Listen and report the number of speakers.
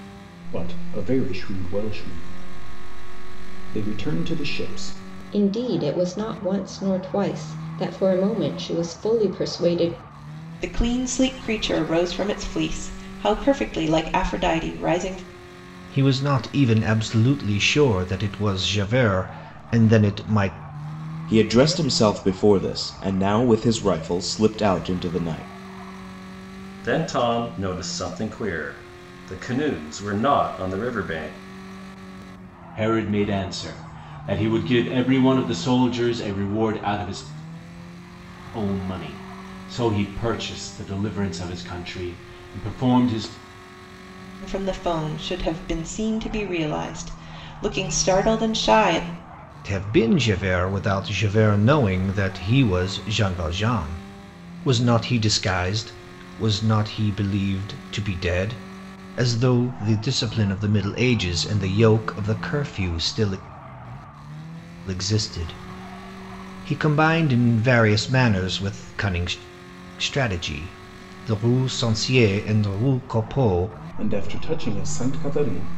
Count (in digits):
7